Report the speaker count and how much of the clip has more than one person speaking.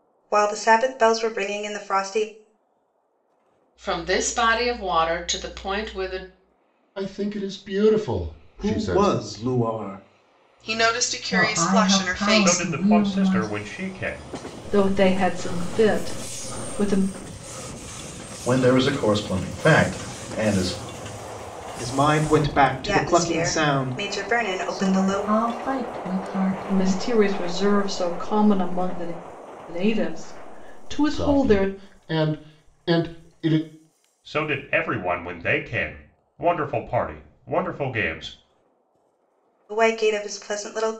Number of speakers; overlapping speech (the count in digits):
9, about 14%